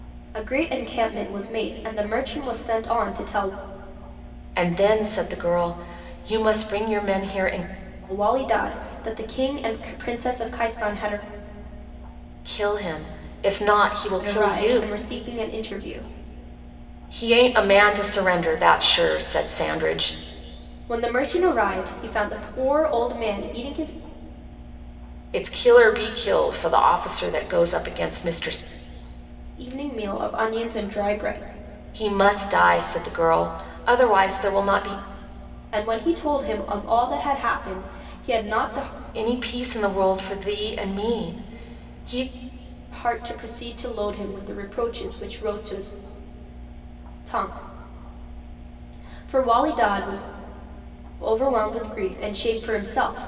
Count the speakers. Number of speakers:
2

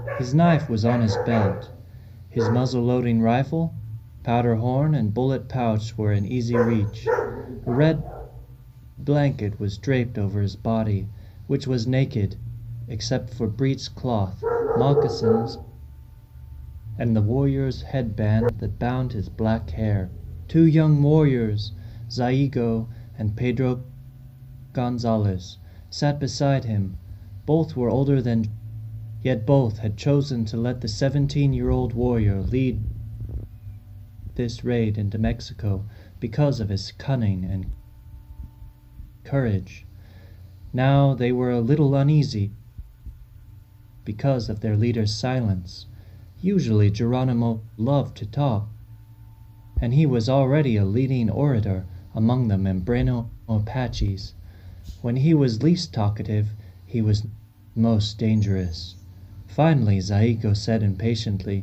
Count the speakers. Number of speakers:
1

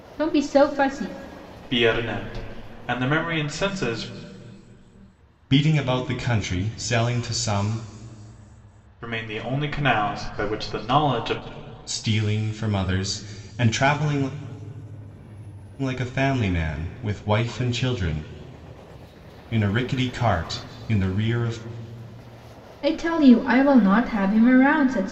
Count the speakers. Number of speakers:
3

